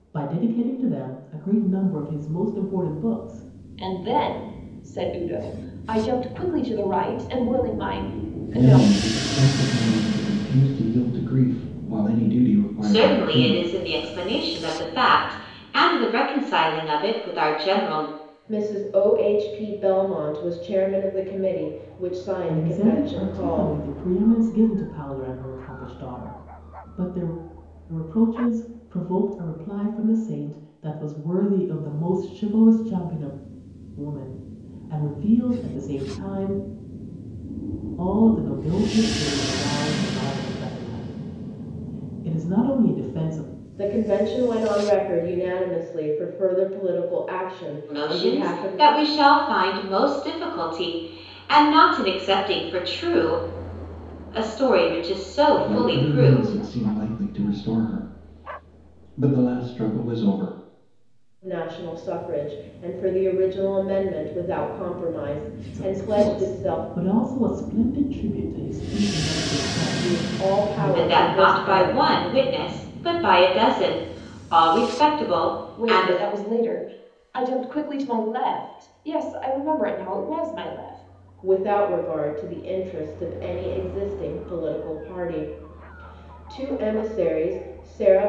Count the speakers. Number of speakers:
5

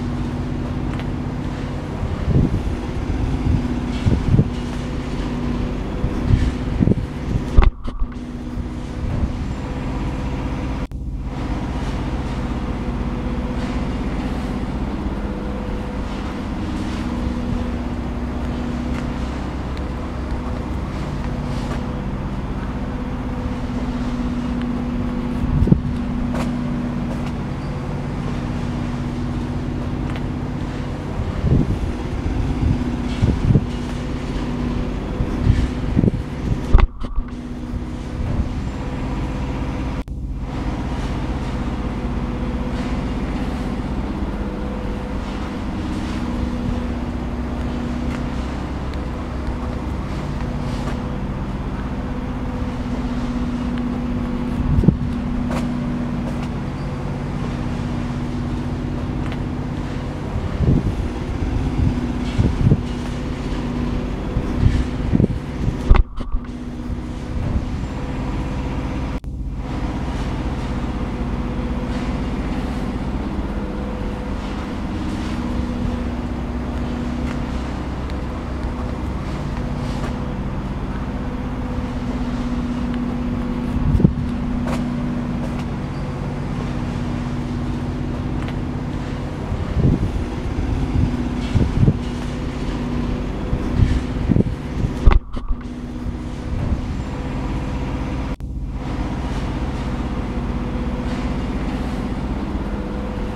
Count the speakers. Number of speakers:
0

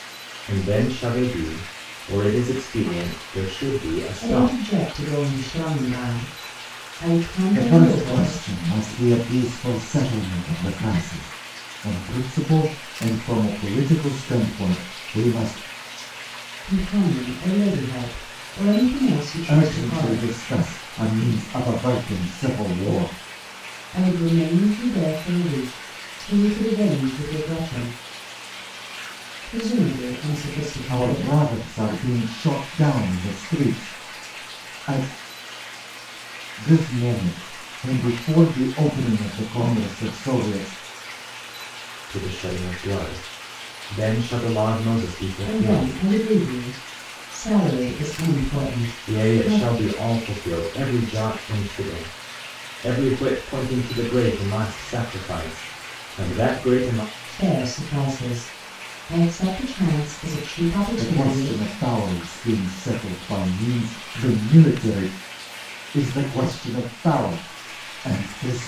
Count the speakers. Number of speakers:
3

